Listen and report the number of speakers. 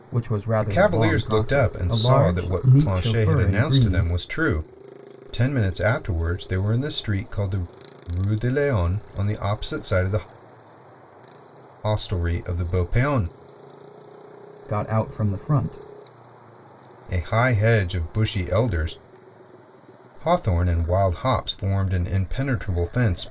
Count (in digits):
2